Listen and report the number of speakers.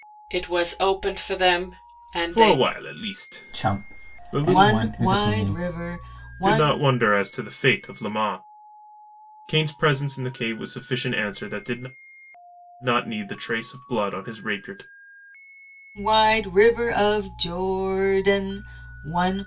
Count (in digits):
4